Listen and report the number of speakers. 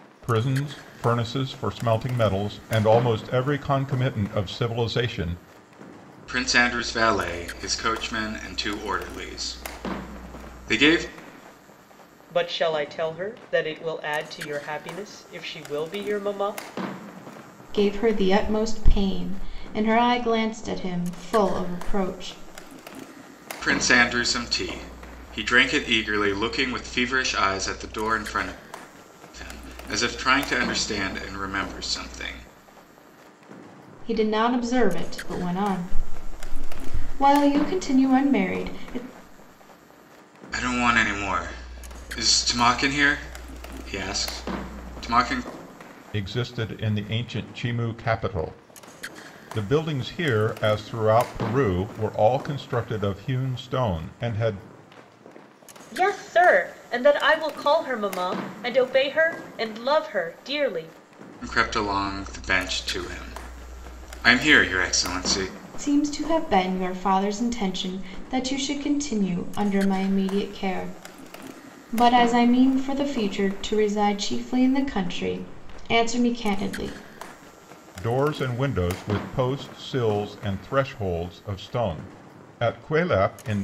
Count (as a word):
four